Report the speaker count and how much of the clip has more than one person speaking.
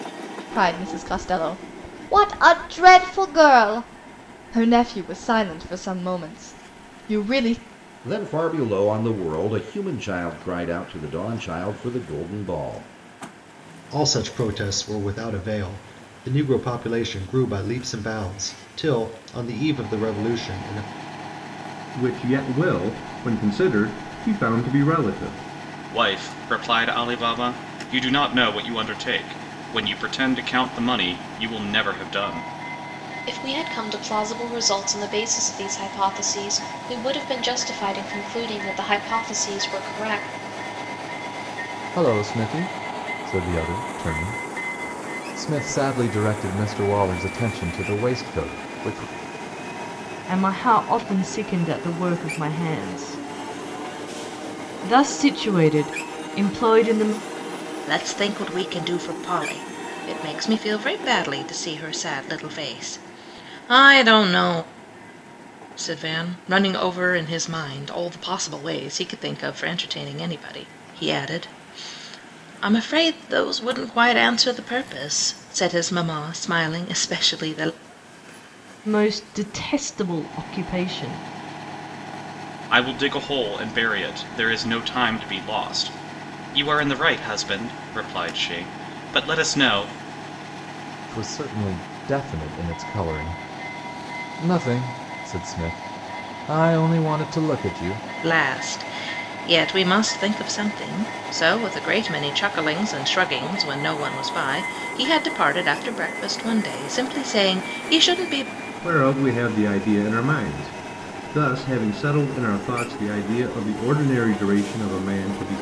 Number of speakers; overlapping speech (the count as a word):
nine, no overlap